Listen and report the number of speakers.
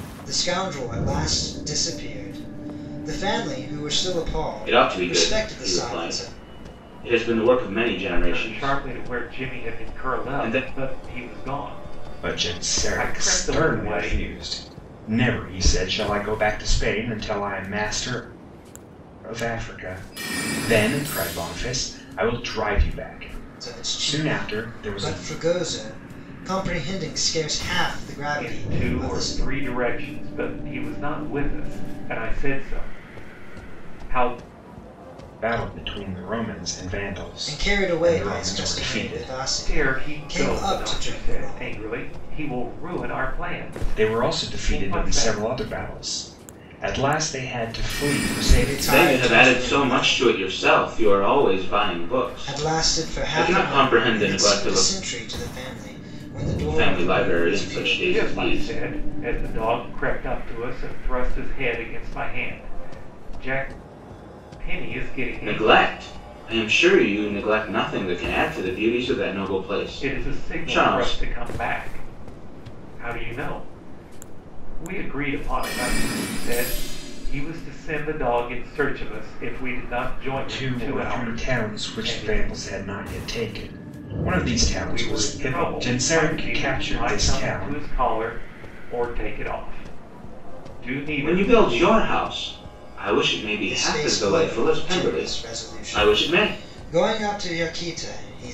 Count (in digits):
4